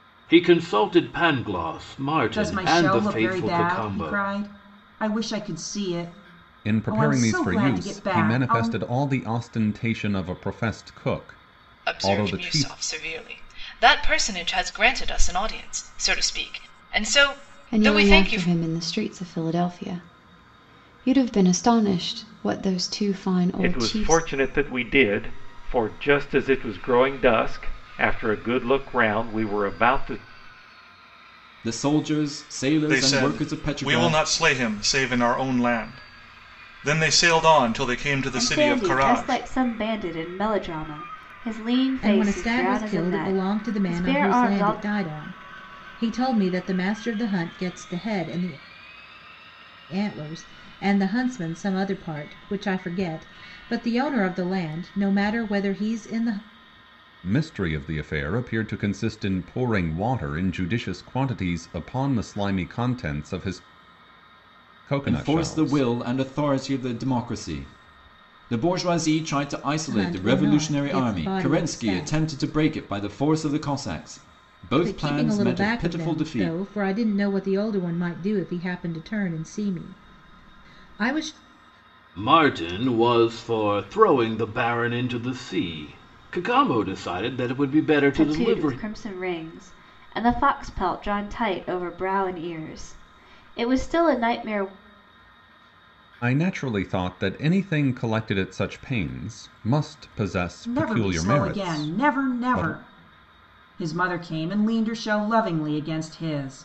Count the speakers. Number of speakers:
ten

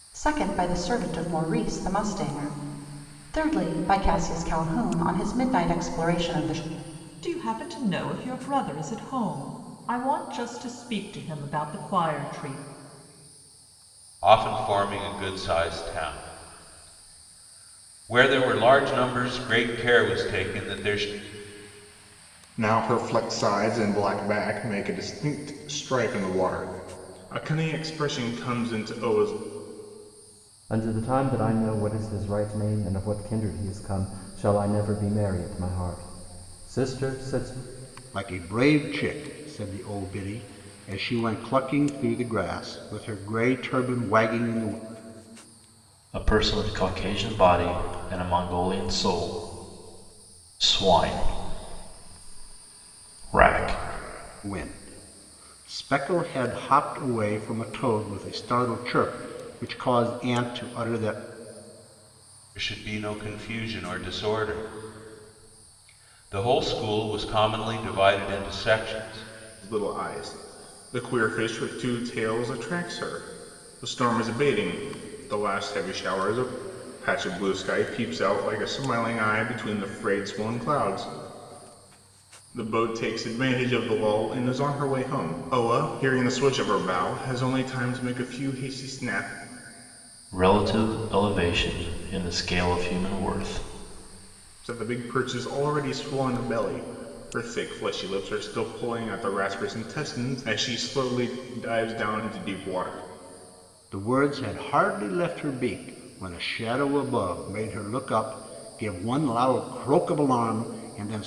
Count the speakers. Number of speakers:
seven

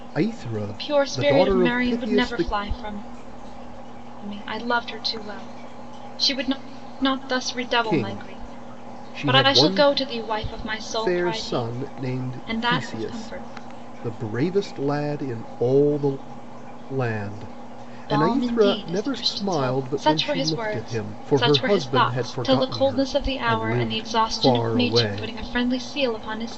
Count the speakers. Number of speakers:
two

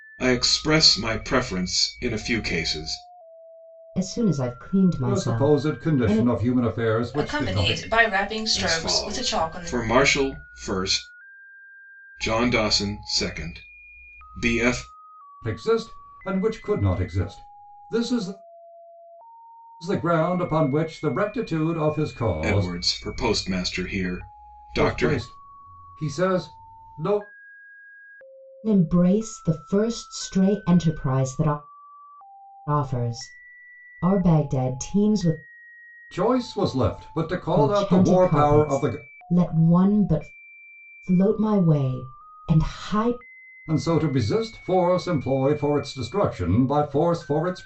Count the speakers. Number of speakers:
four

